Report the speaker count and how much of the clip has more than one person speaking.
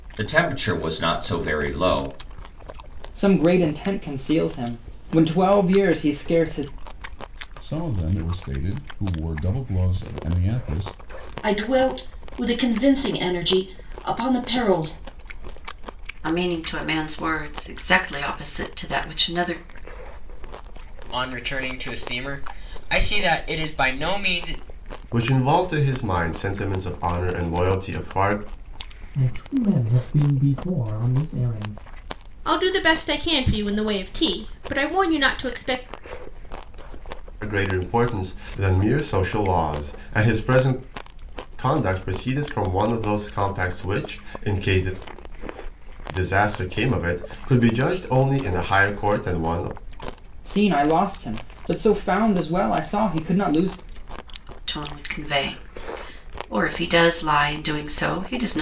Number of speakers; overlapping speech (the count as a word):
nine, no overlap